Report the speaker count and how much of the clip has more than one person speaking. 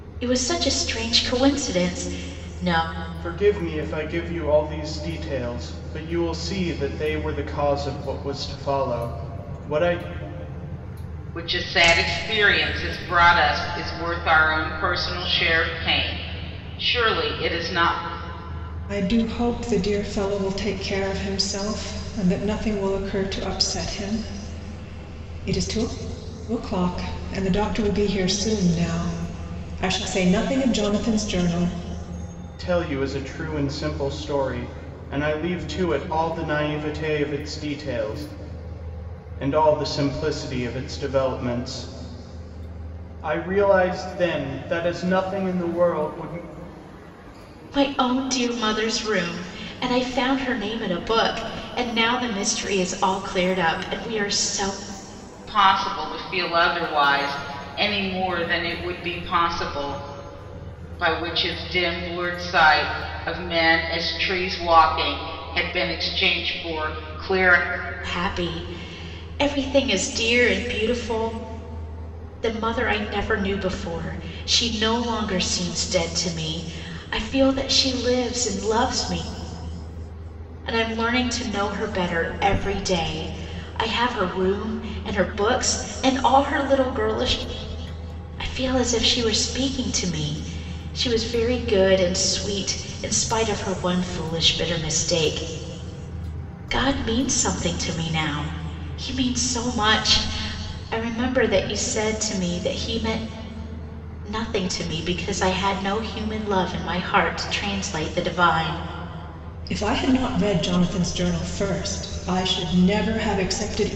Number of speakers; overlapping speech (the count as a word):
four, no overlap